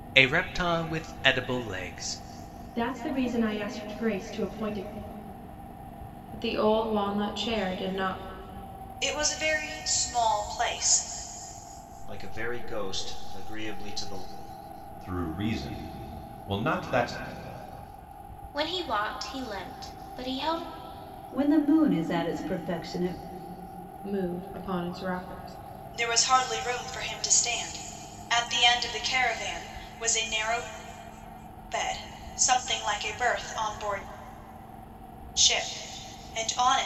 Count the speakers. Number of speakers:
8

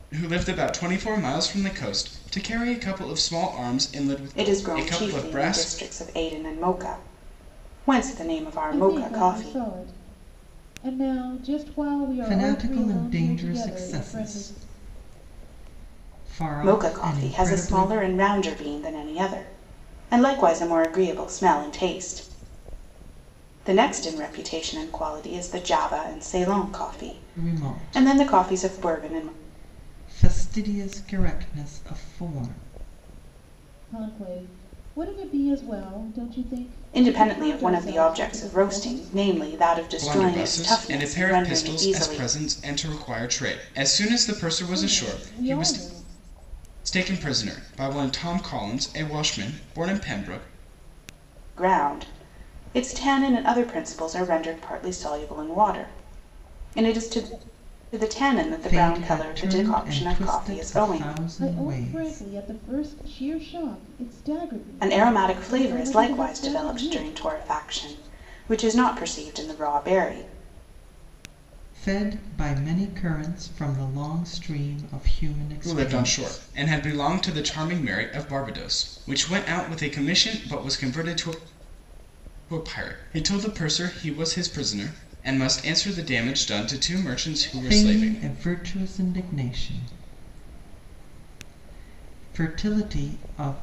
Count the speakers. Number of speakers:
4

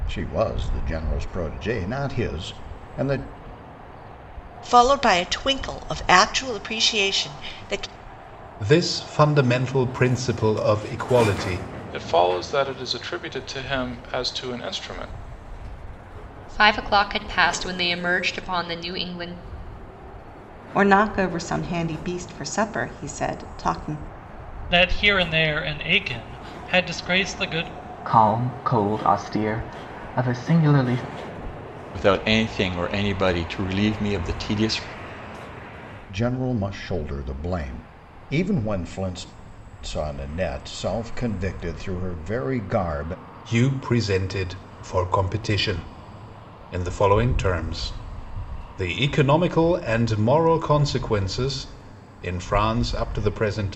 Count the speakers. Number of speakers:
9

